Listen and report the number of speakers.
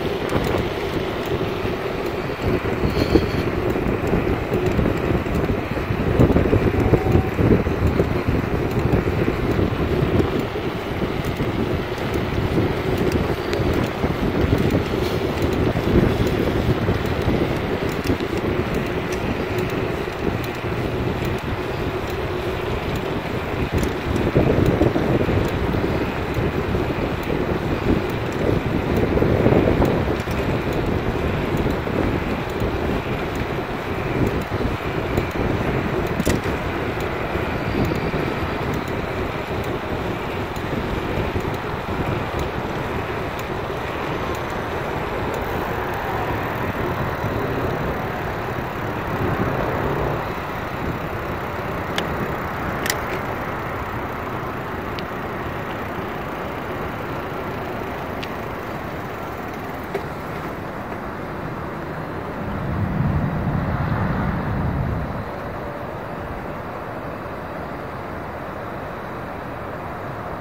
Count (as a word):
zero